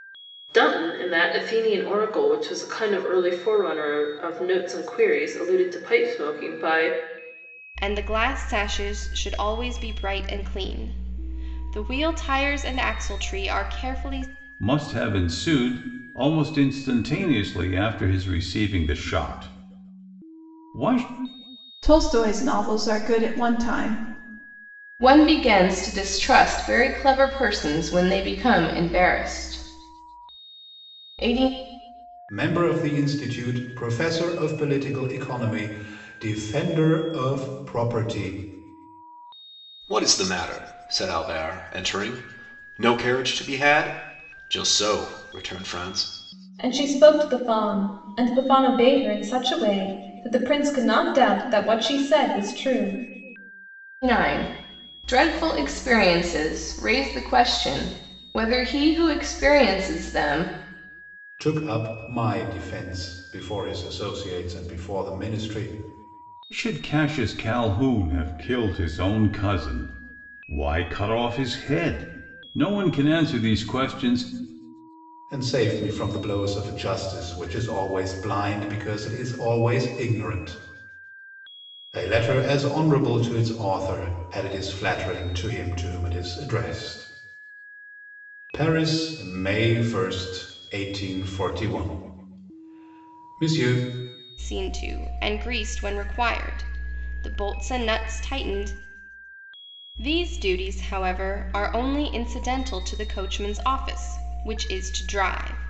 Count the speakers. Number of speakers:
eight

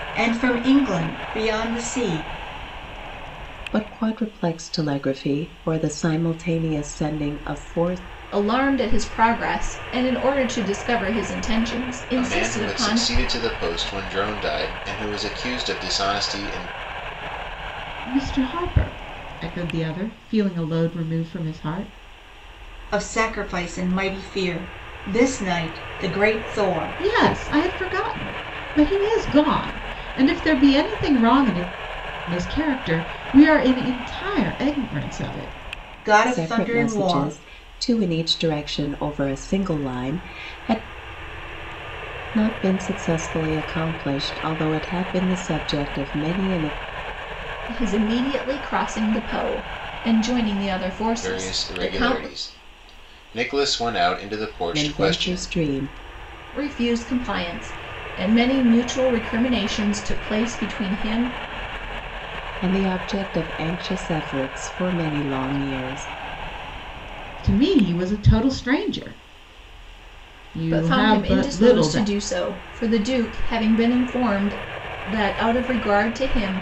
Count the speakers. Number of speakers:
five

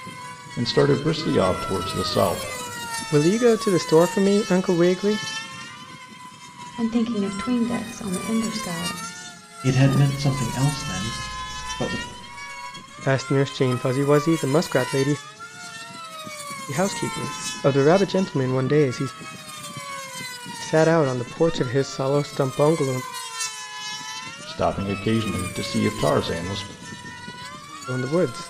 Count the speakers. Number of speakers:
four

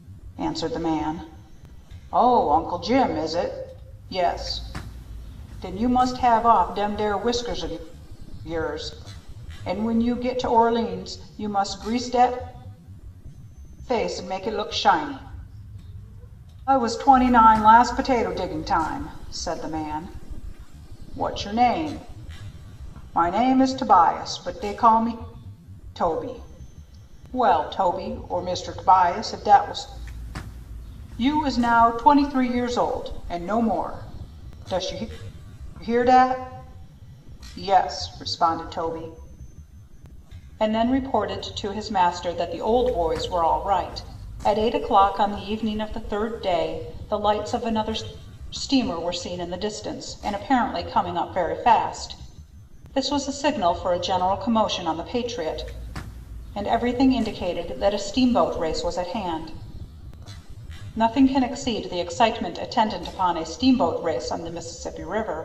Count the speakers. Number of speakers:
one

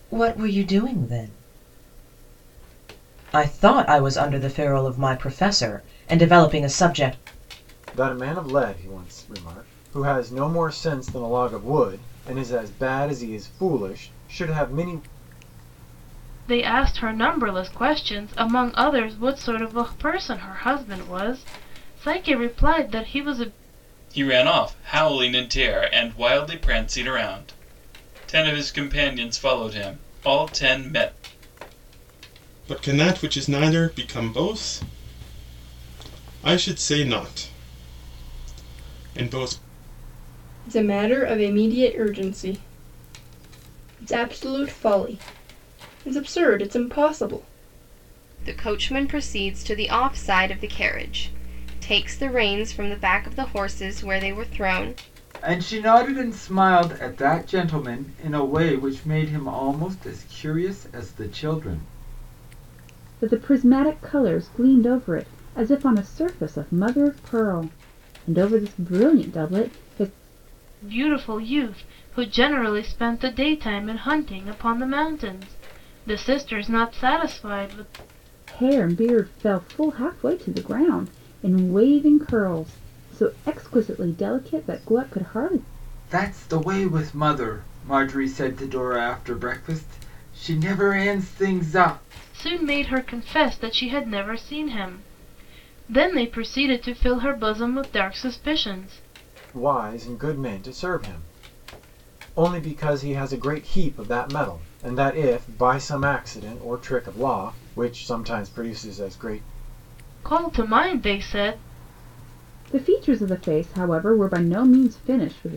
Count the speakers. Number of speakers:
nine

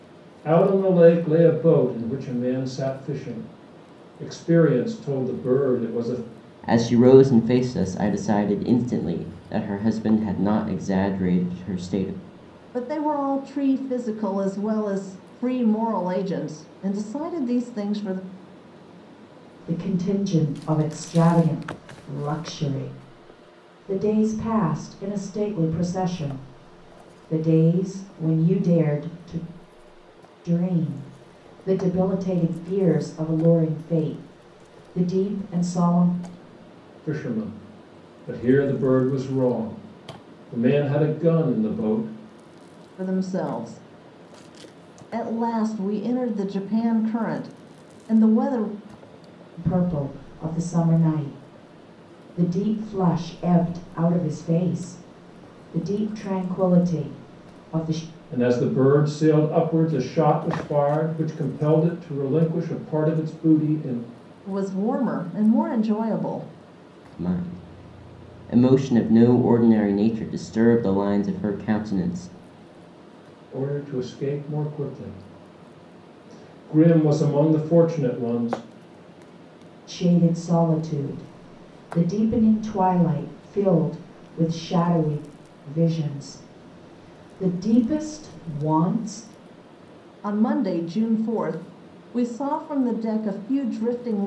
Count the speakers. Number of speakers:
four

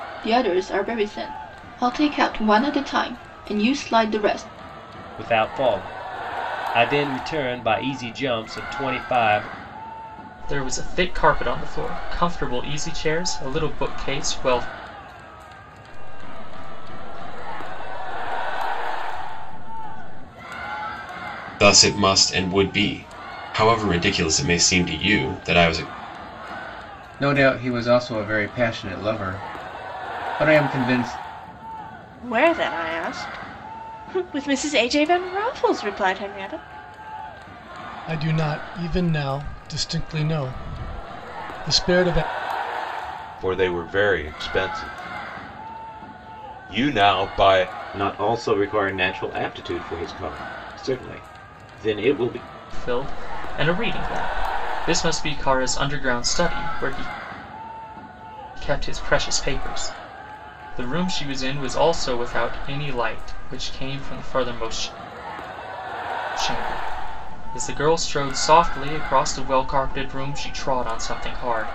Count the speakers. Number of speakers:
ten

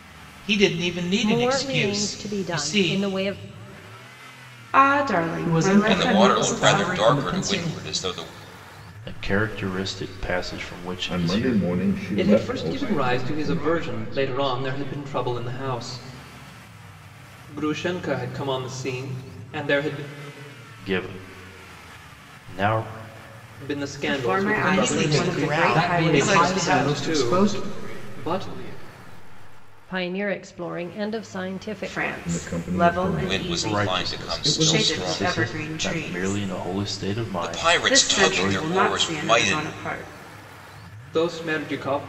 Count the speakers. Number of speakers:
nine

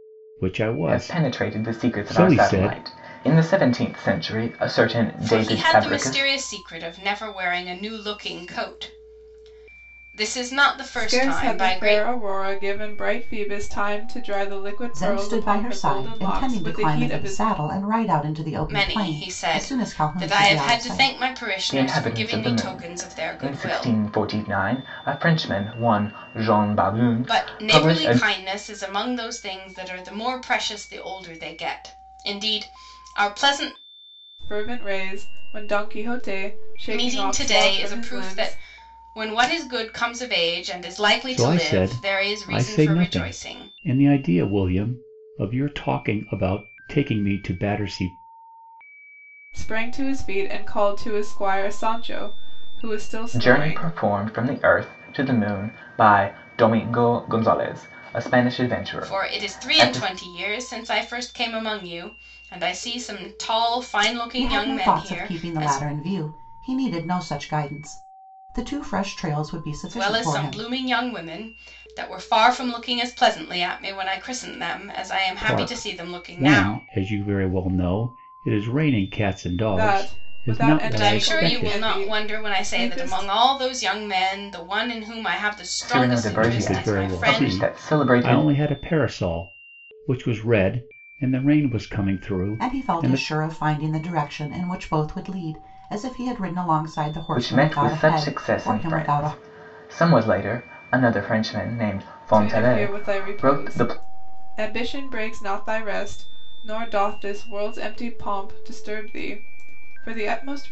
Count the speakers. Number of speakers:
five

